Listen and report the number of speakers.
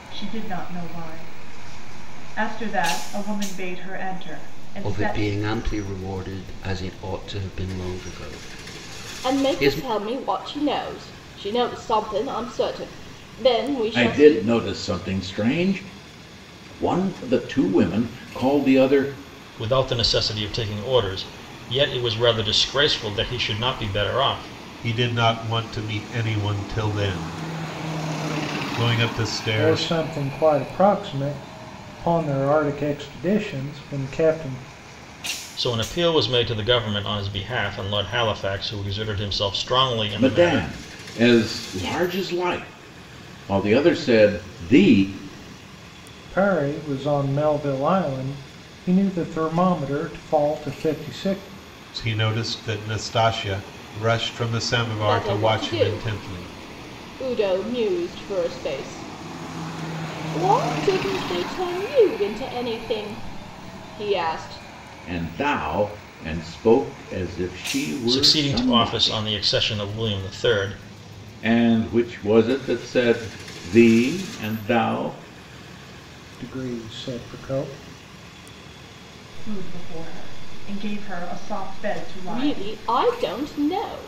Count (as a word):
seven